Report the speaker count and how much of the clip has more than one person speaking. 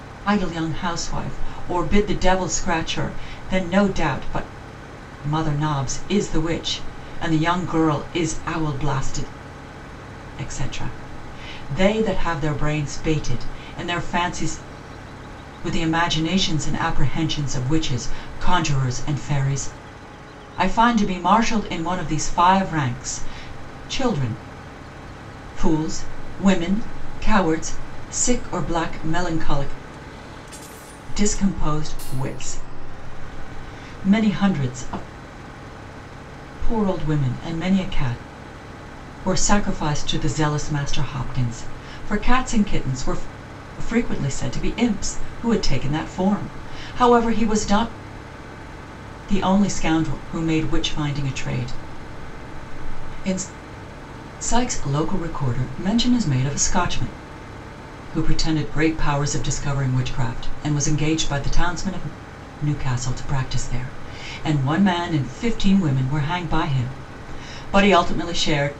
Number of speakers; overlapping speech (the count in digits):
1, no overlap